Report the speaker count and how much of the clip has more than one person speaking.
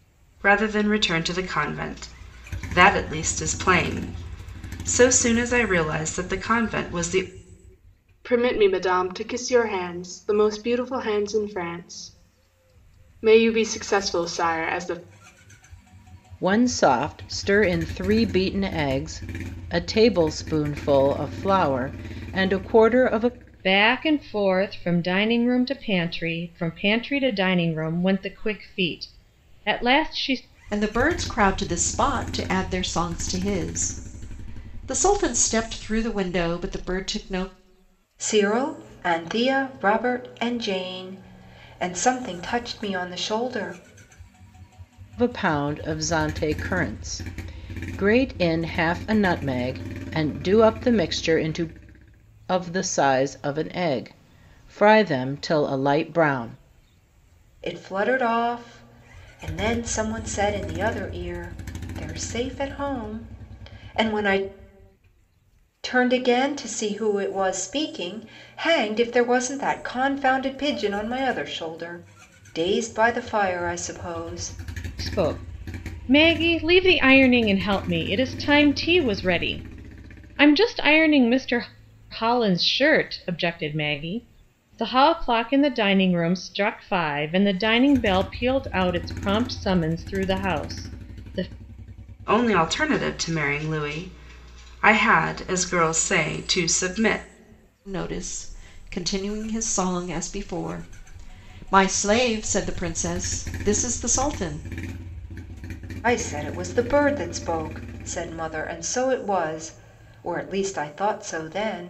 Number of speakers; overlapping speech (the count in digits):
6, no overlap